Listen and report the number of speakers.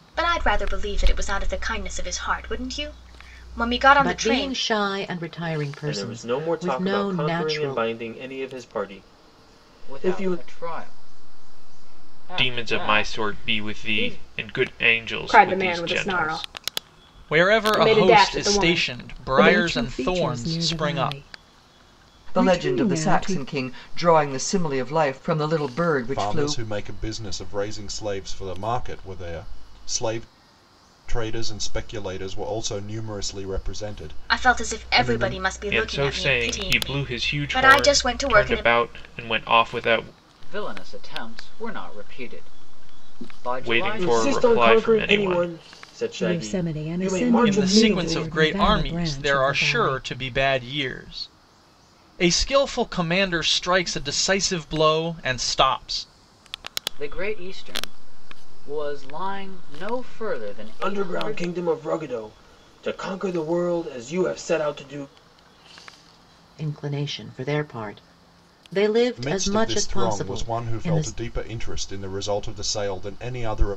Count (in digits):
10